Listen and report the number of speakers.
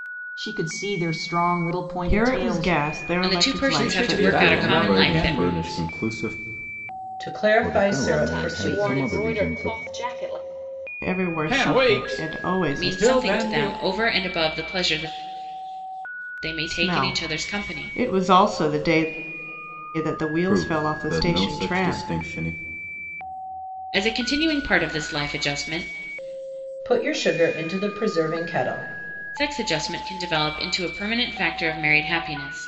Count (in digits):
8